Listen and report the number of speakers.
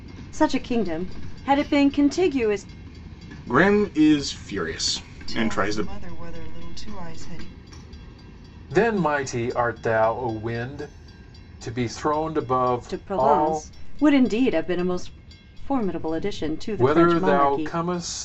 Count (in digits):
4